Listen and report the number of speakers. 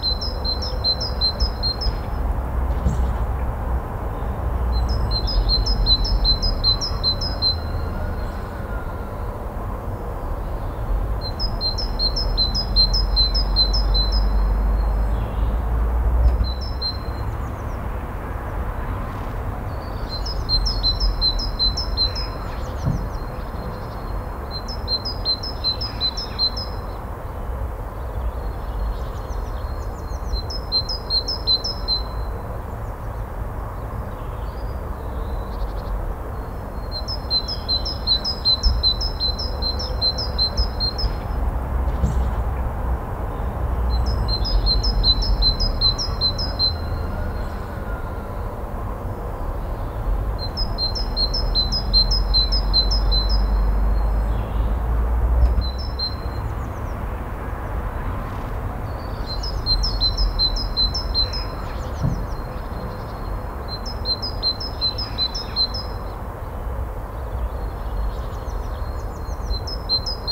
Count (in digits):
0